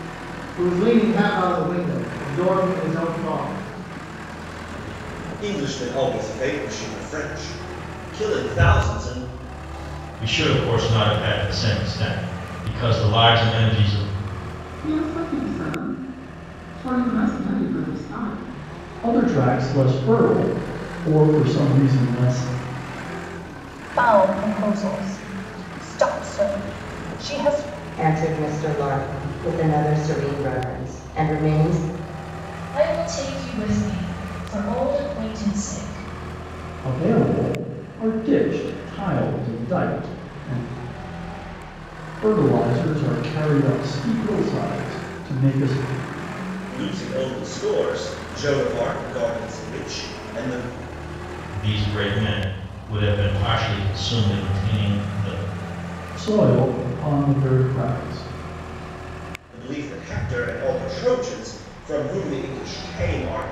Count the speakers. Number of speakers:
eight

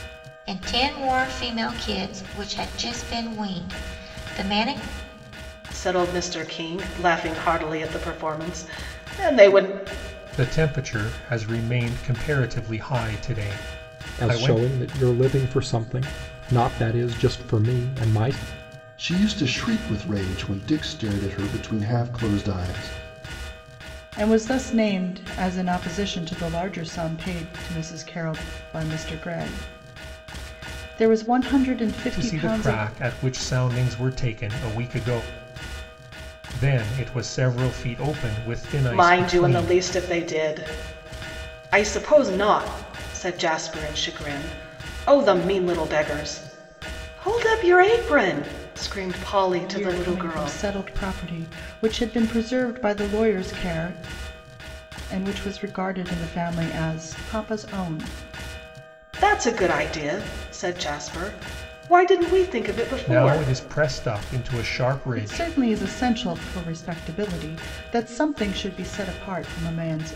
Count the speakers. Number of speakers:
six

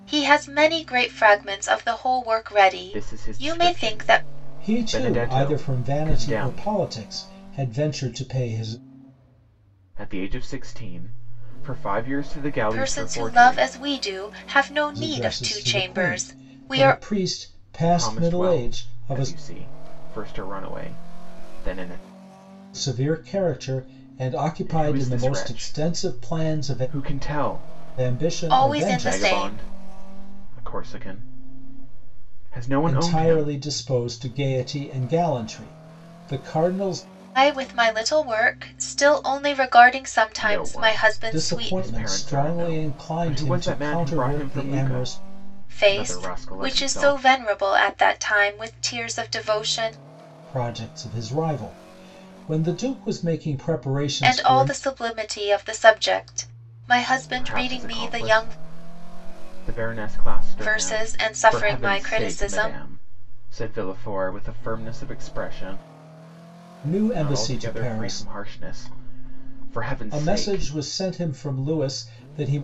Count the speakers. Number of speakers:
three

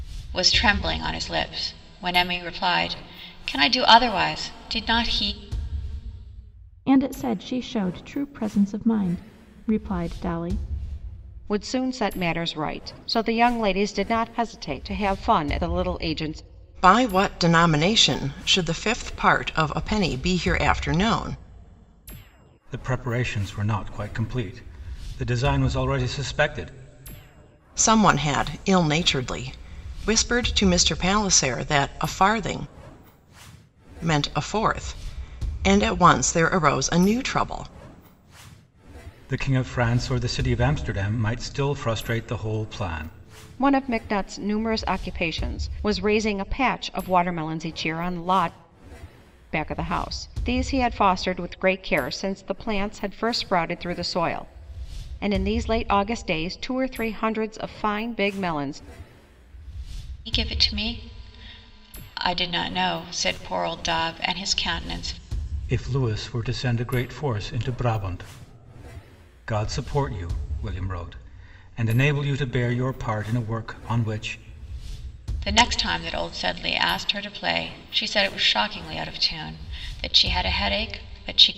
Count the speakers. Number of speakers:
five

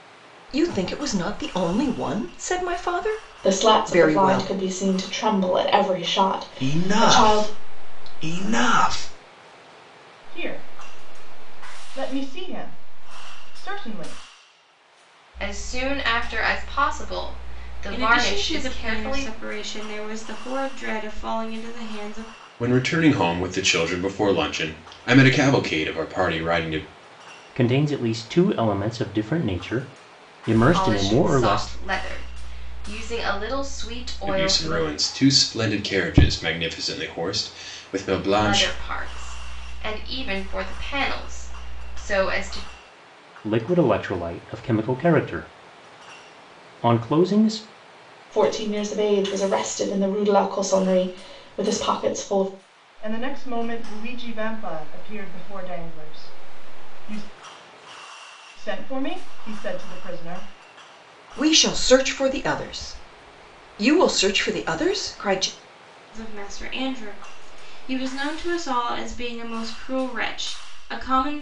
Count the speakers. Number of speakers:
eight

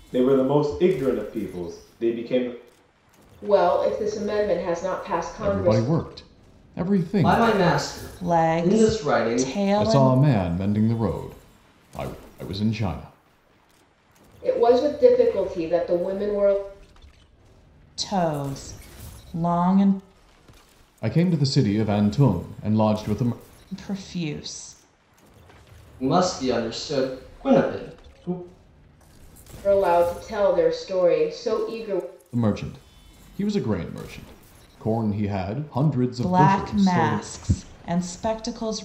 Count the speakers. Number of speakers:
five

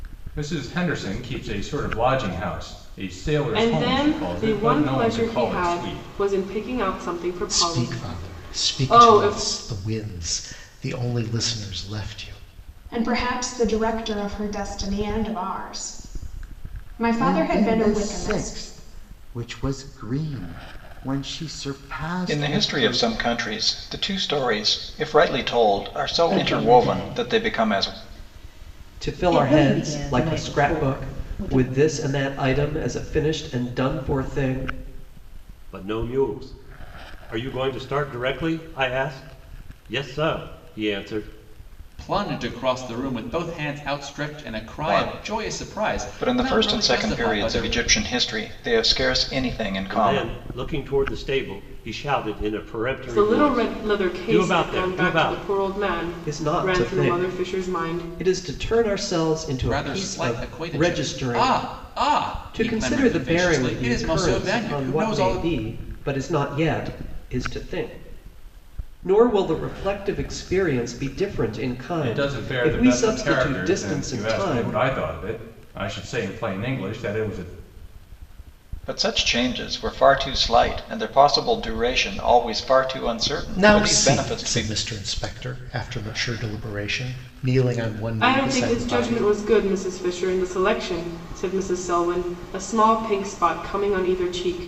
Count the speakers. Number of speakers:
ten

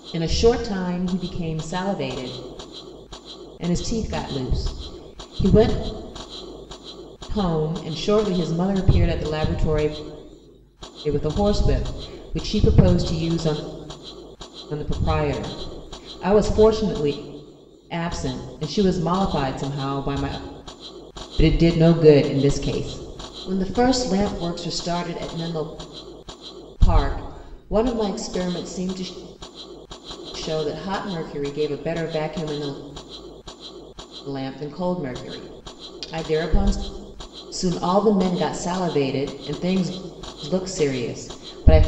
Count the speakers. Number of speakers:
one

